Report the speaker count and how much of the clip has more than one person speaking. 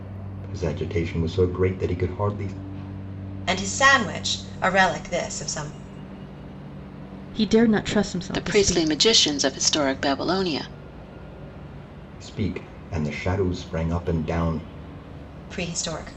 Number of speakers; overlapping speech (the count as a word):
four, about 4%